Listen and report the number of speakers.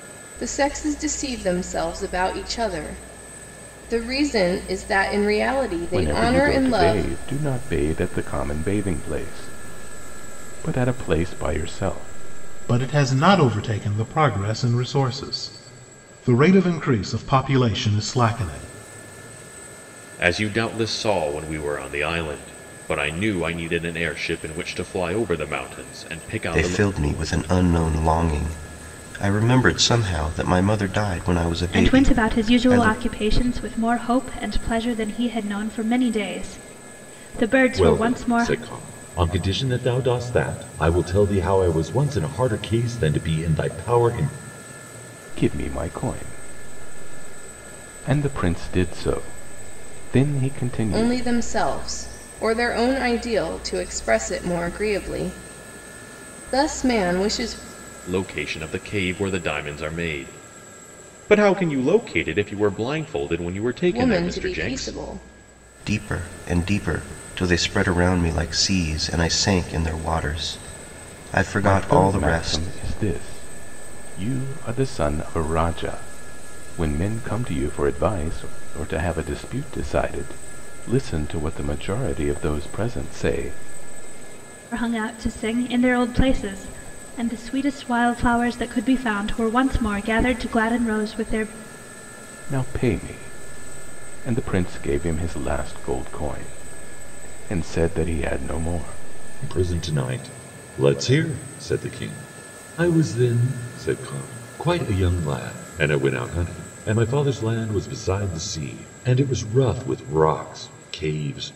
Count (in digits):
7